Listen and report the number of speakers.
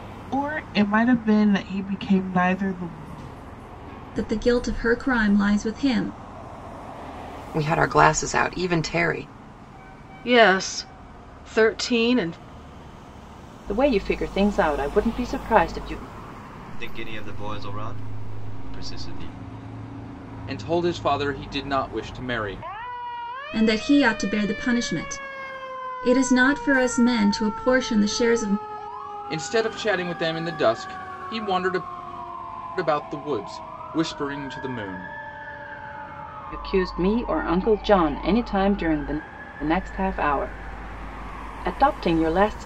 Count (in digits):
7